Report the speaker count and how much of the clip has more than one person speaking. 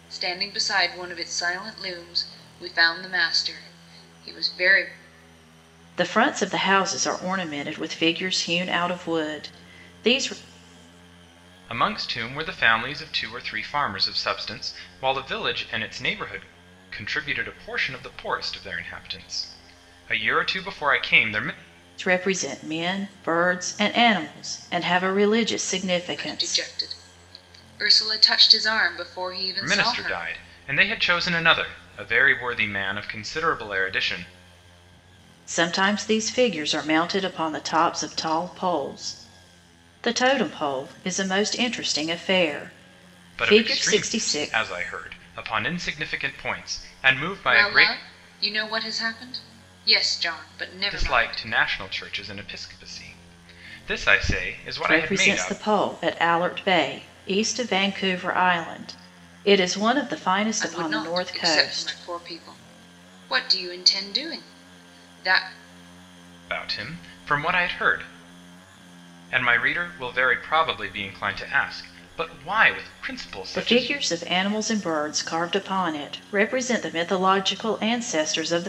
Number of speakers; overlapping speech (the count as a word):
three, about 8%